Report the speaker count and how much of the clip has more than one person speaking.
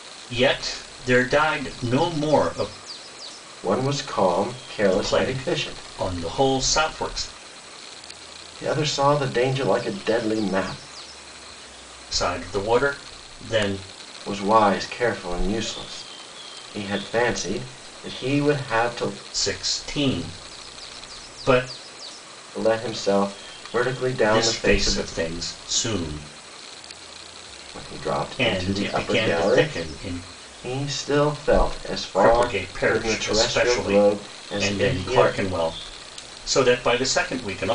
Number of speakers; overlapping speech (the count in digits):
2, about 16%